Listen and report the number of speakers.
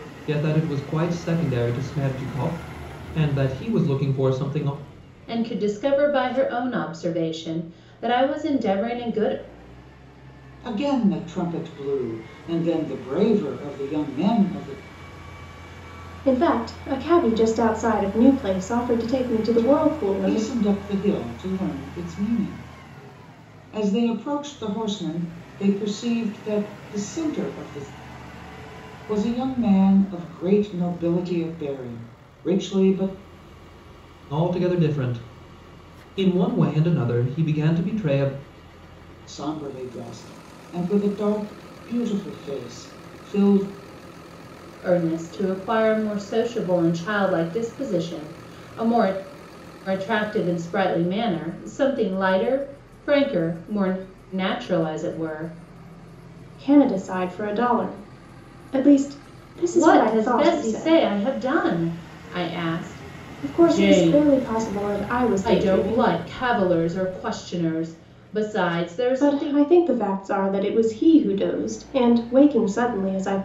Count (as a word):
four